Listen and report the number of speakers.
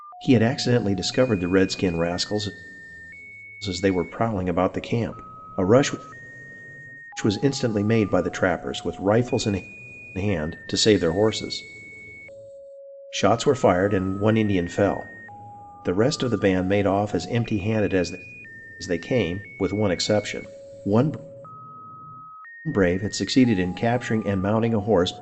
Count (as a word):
one